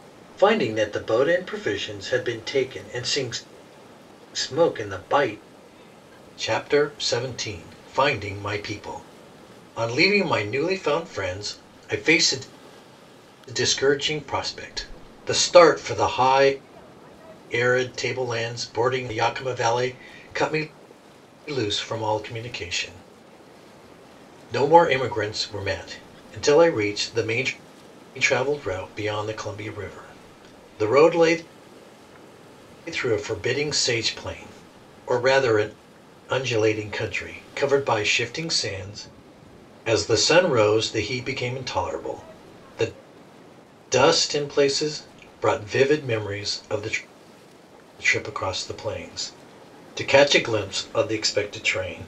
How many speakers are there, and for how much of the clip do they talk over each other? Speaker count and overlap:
one, no overlap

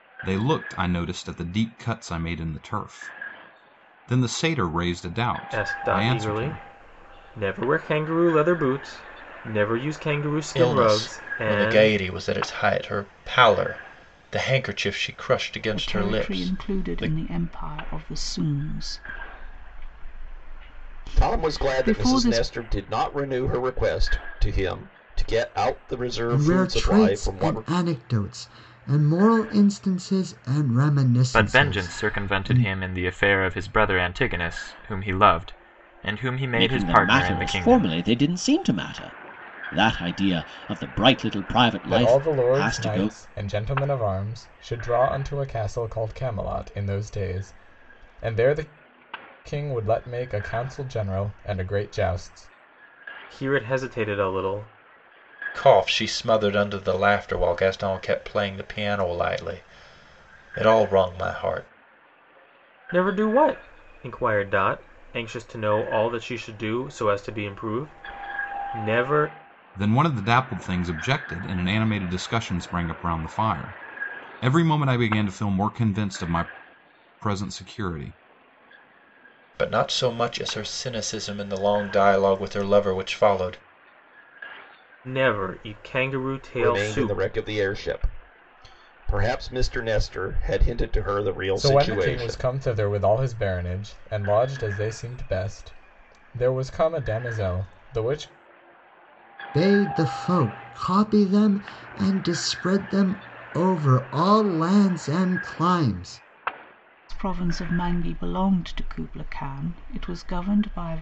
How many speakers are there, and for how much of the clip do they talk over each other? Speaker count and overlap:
nine, about 11%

